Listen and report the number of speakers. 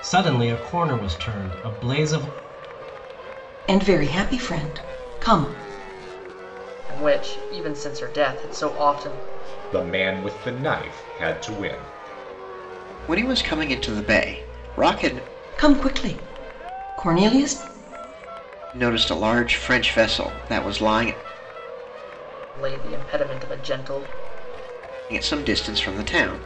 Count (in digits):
5